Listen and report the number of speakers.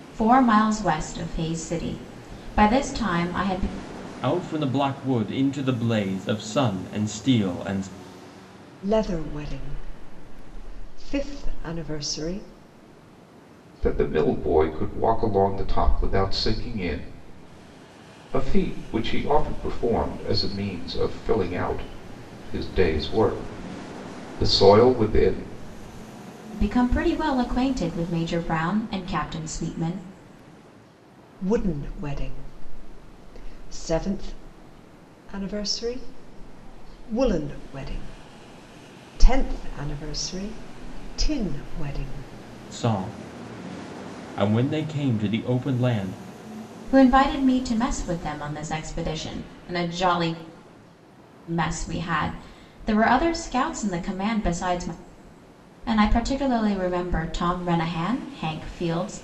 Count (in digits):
4